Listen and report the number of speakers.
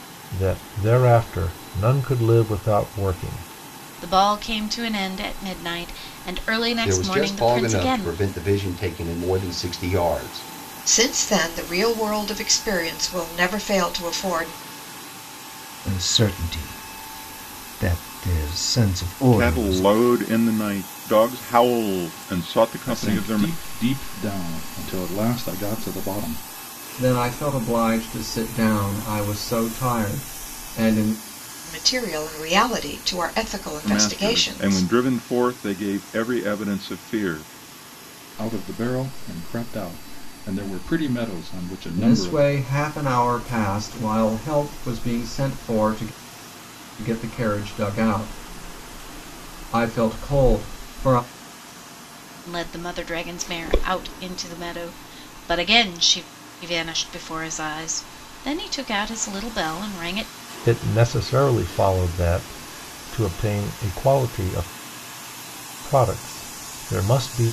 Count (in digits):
8